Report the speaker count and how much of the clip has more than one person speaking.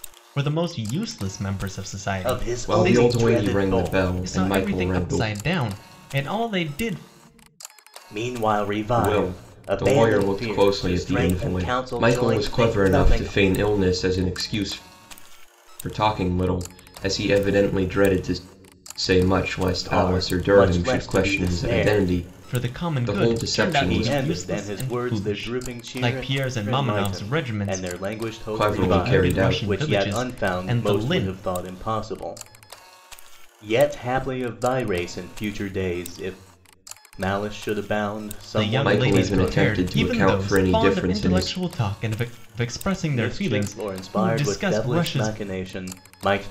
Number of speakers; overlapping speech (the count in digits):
3, about 49%